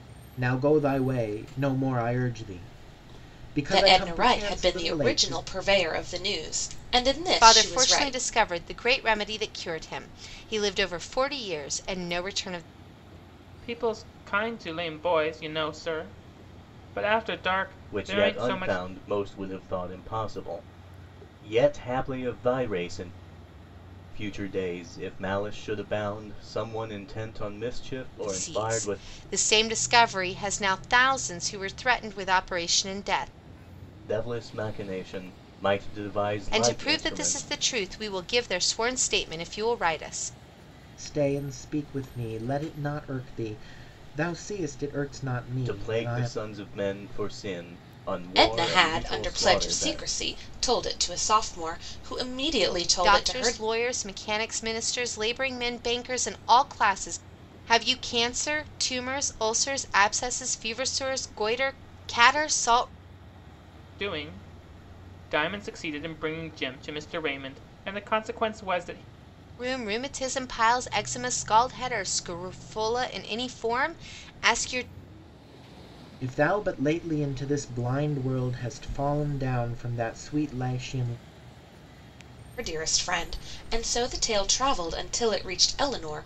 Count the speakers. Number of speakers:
five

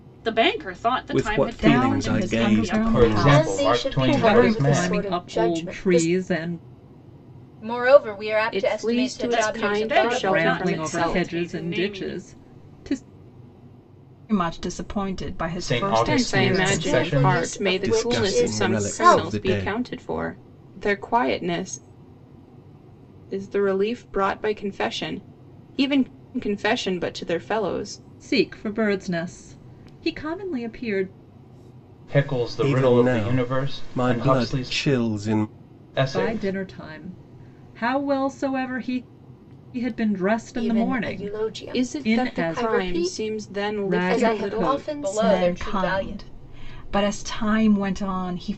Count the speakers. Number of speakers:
eight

